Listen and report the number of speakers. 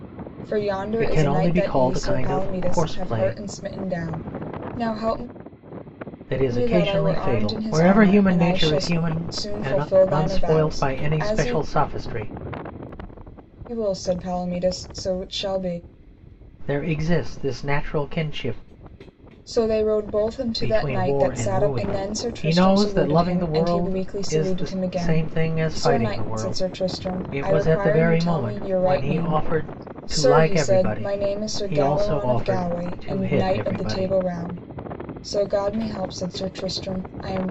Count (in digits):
2